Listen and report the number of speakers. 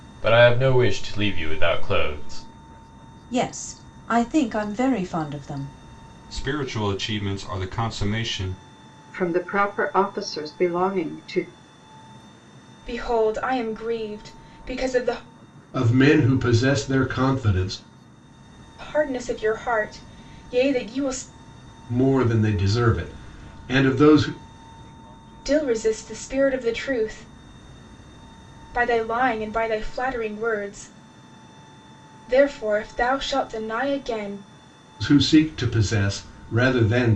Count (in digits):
6